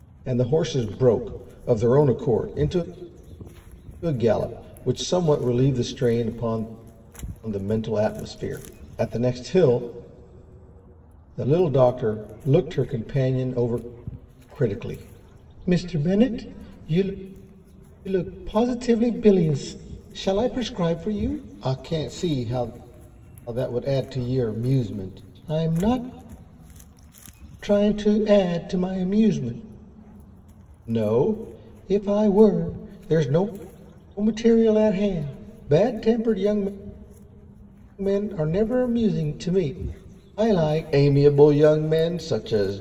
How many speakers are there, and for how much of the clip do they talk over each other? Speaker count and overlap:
1, no overlap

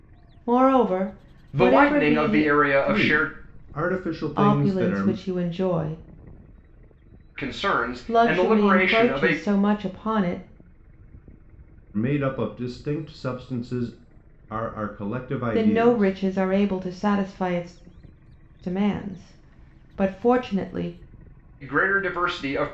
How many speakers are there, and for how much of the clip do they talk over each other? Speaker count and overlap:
3, about 19%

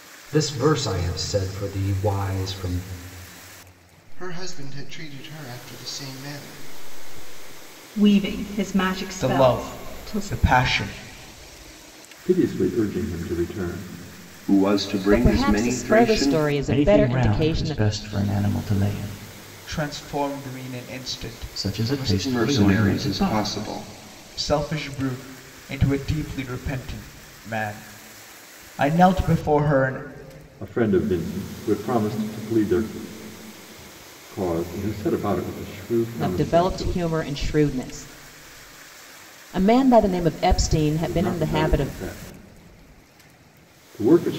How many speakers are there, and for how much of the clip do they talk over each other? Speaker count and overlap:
8, about 17%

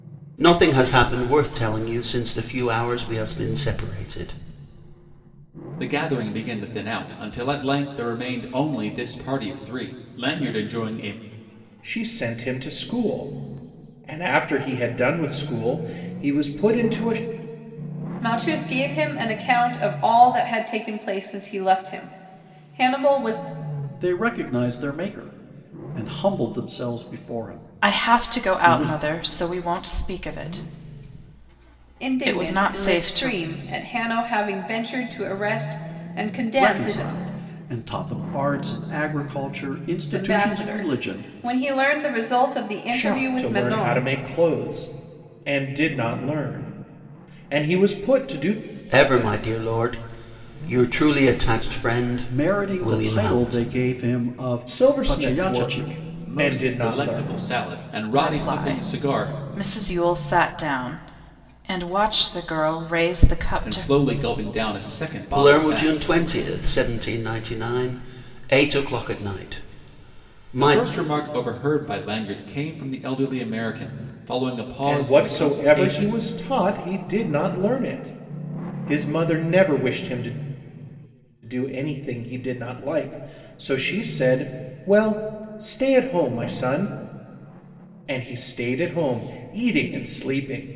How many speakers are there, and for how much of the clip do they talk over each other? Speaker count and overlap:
6, about 15%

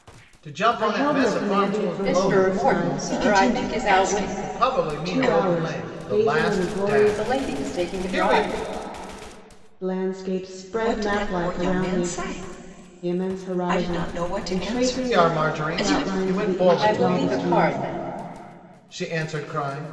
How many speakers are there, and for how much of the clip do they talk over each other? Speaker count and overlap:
4, about 66%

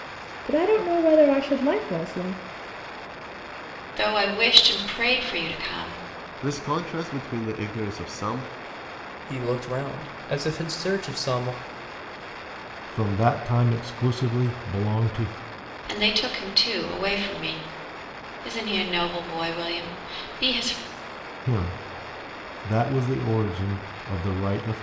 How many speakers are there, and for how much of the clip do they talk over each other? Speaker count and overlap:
5, no overlap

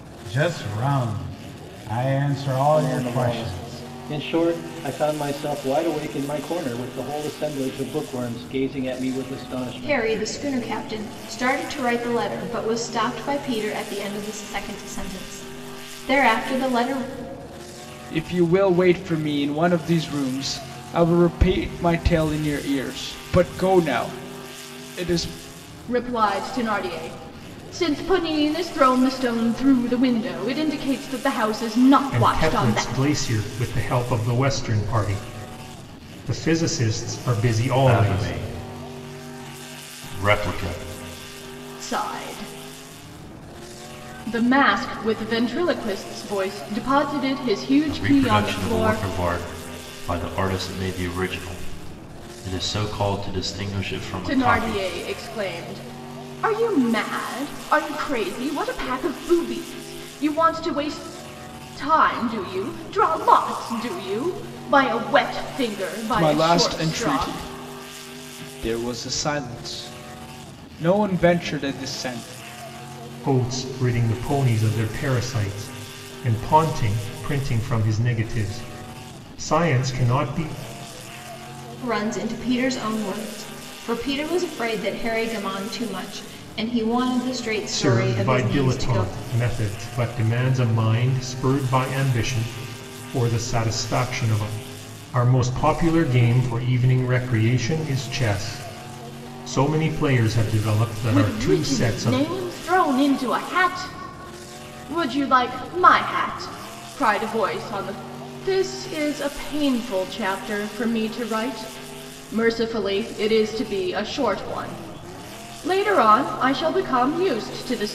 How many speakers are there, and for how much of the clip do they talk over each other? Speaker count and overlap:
7, about 7%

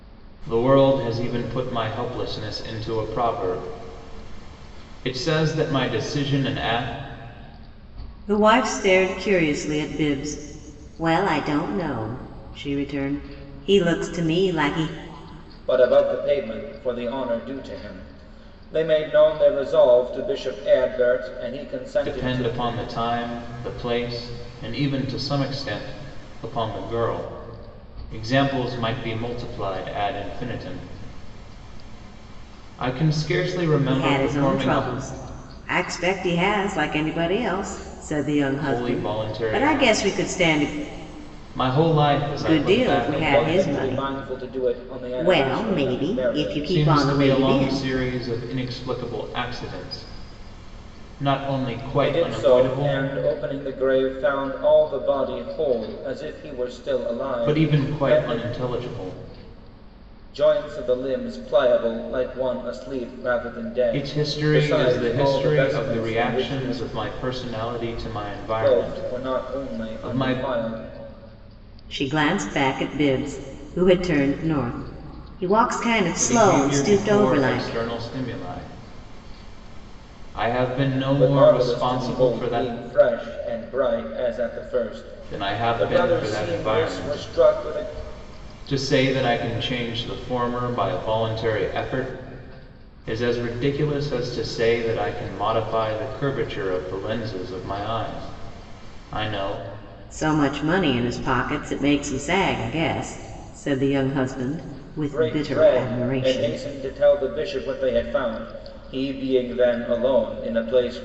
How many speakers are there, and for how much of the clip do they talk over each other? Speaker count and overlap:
3, about 20%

